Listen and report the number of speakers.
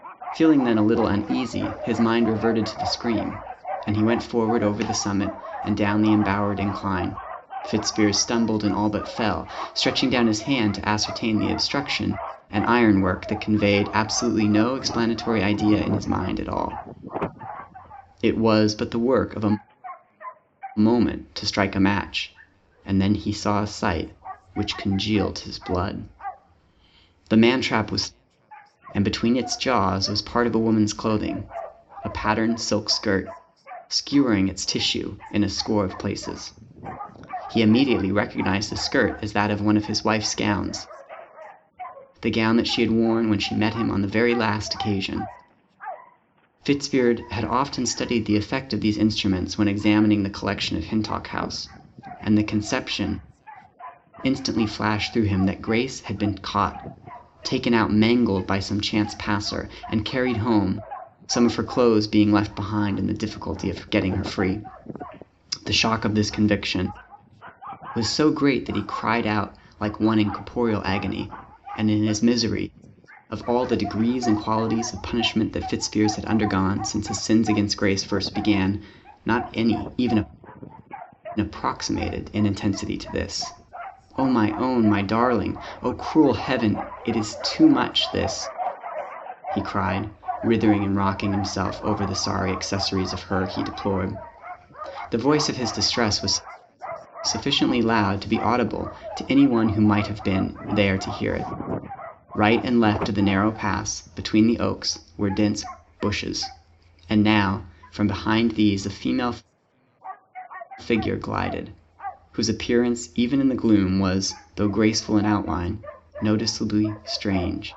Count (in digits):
1